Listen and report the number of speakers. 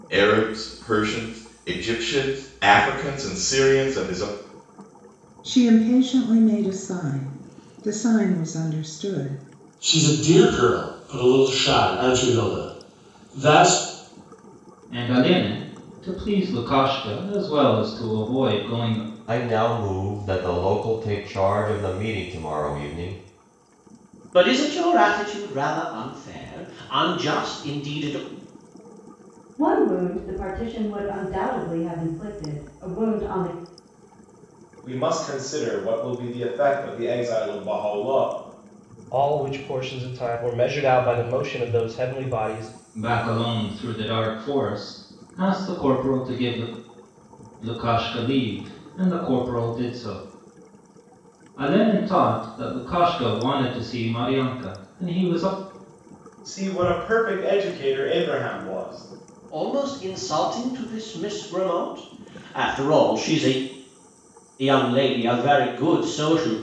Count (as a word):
nine